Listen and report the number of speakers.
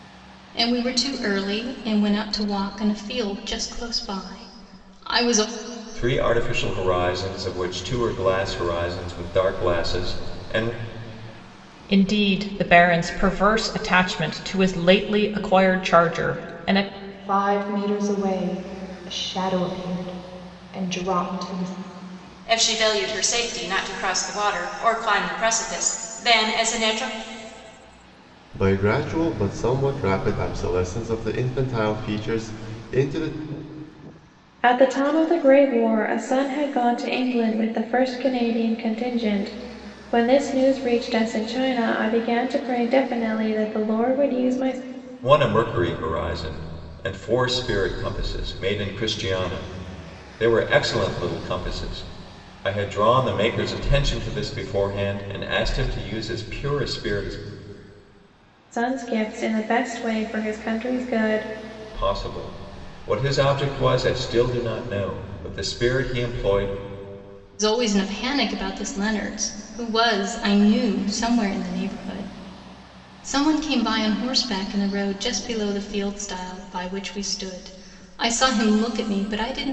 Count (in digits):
7